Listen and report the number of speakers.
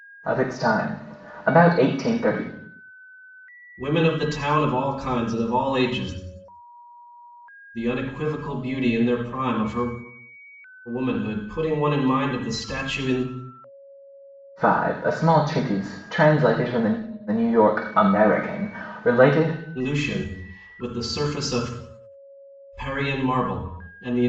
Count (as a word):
two